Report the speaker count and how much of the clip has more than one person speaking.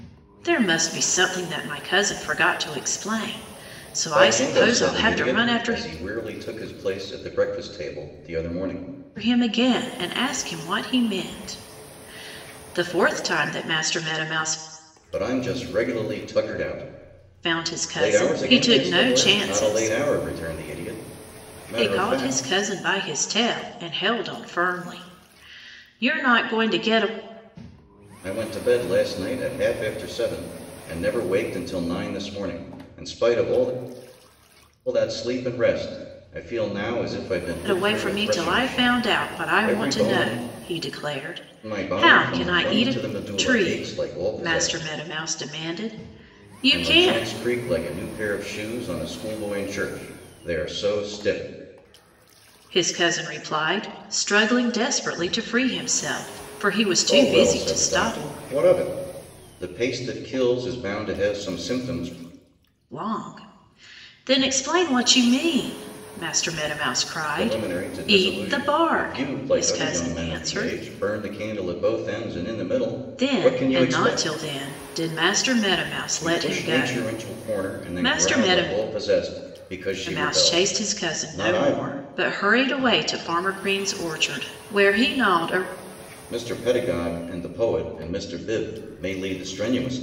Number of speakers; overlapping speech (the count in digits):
2, about 24%